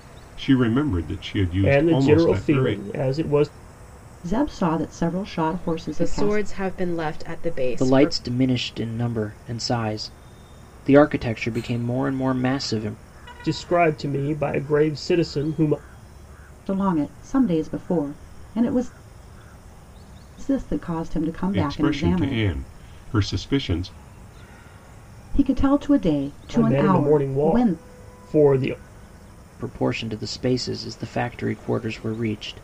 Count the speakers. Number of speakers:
five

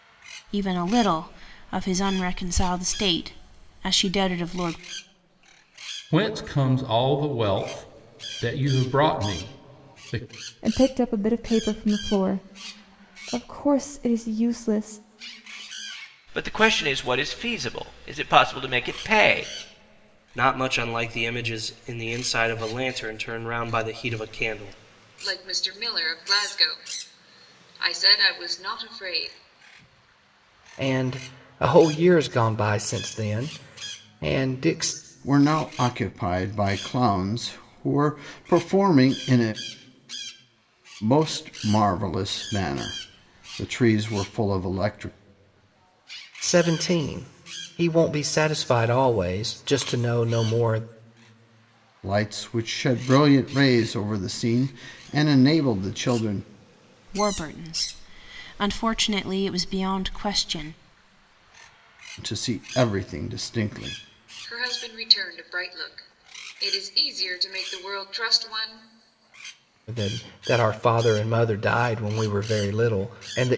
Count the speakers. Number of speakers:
eight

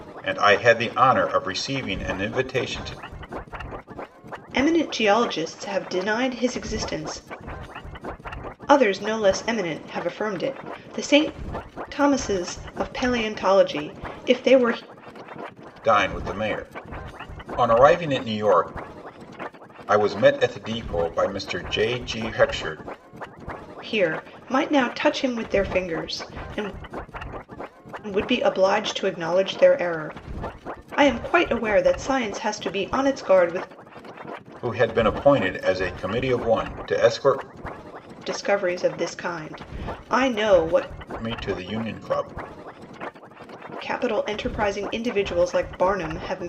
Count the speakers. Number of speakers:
two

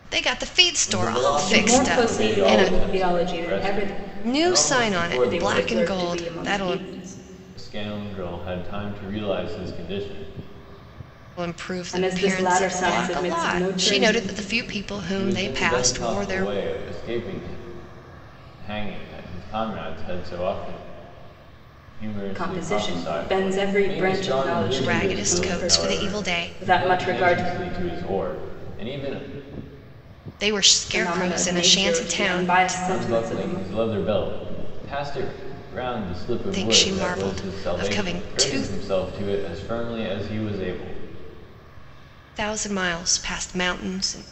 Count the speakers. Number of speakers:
three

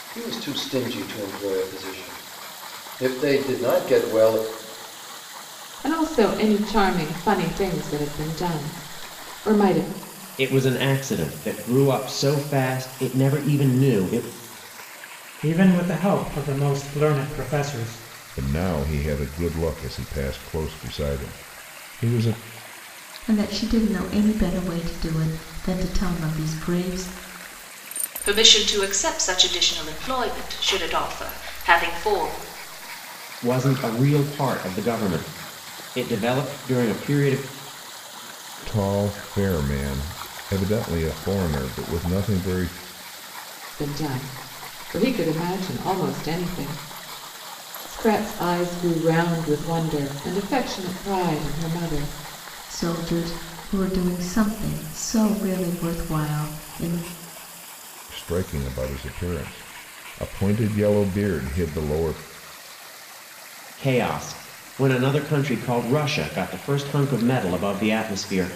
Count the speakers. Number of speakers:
seven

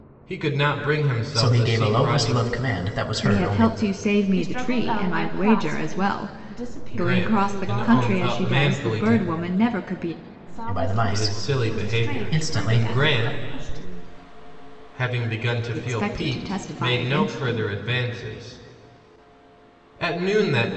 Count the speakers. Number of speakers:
four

